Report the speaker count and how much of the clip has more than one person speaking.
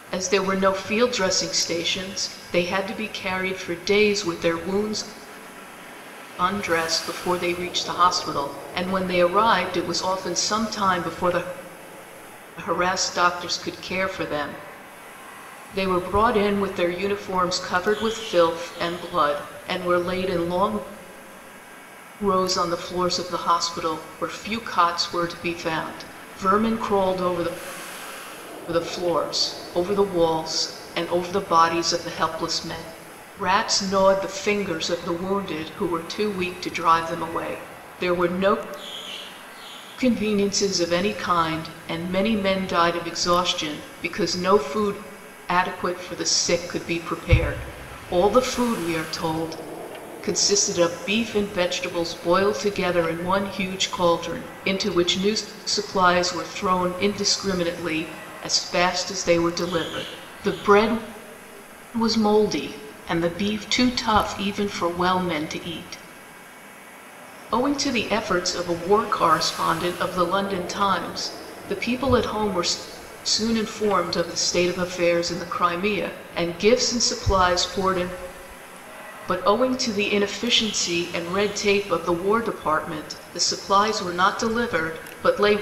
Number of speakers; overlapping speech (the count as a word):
one, no overlap